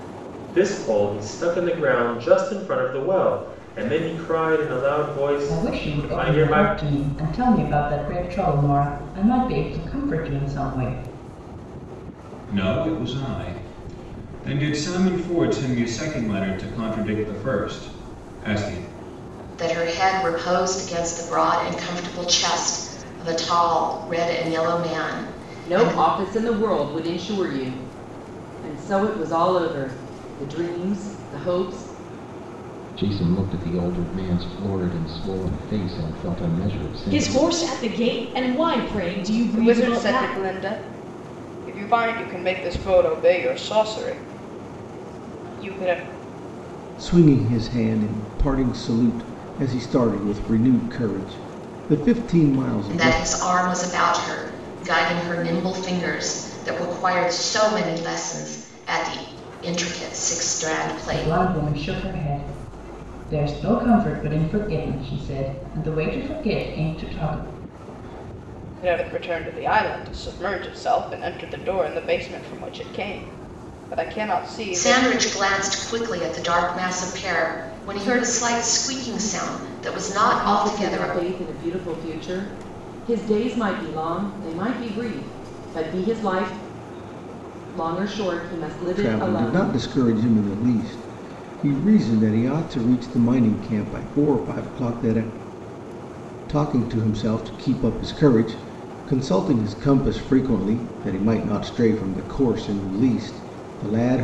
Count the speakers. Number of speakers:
9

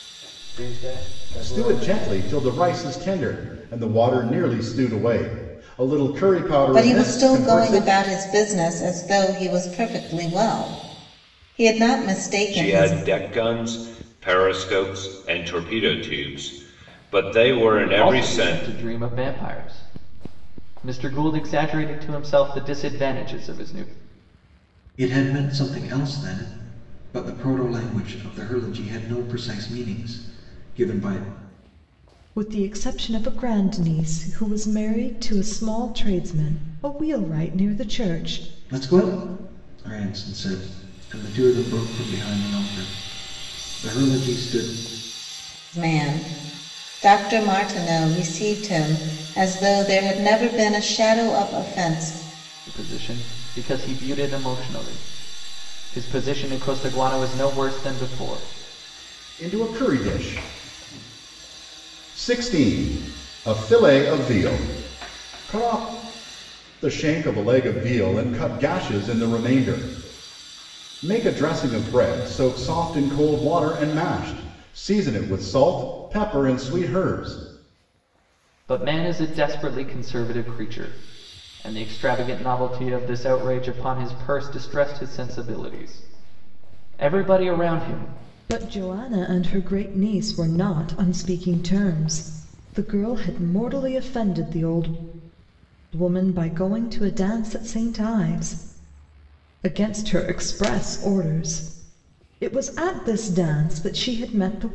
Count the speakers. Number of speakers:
7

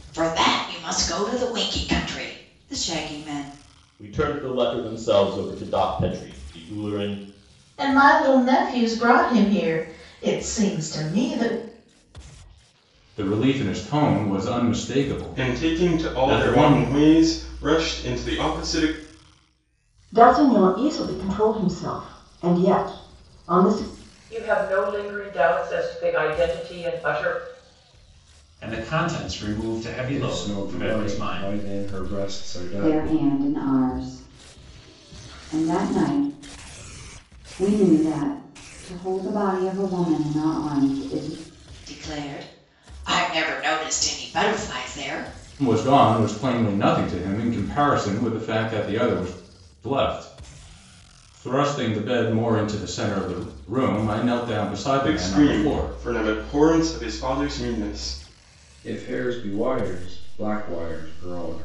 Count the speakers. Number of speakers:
10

